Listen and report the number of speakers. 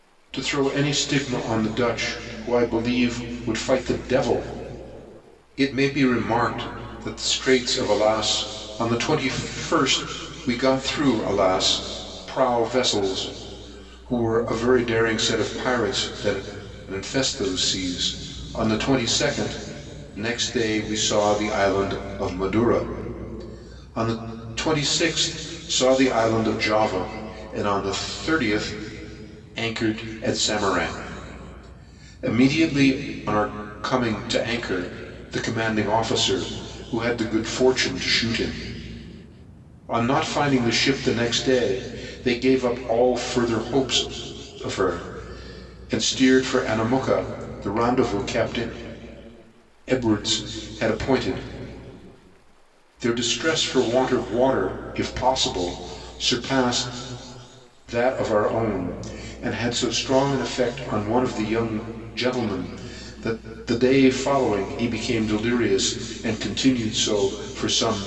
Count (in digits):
1